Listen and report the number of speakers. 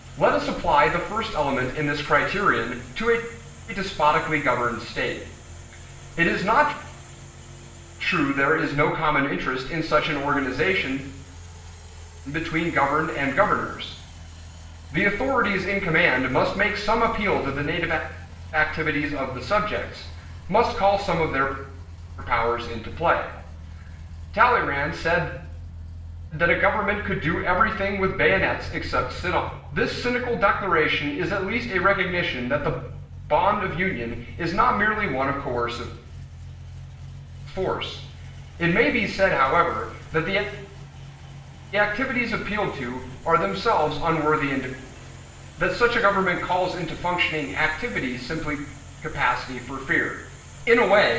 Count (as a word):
one